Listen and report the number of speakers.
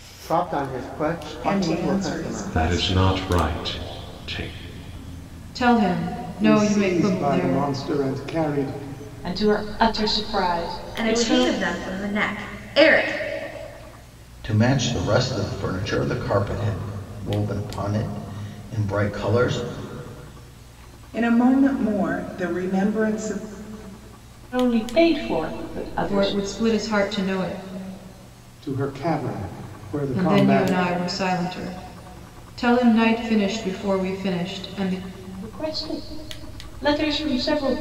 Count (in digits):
8